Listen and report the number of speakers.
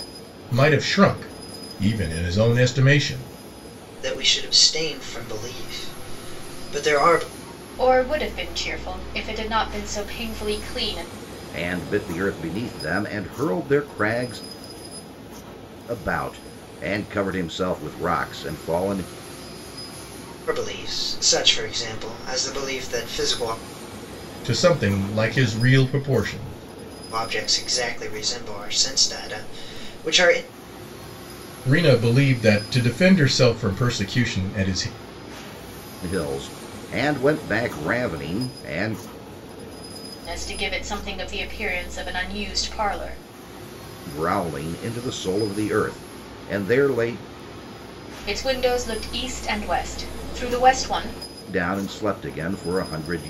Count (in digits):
4